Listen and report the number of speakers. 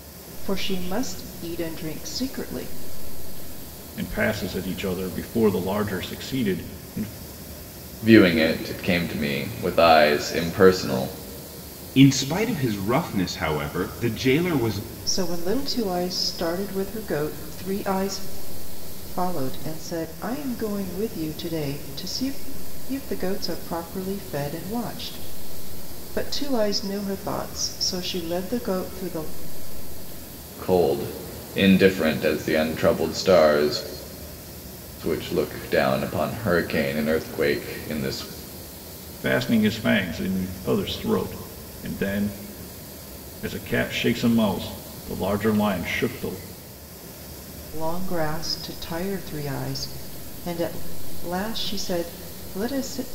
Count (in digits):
4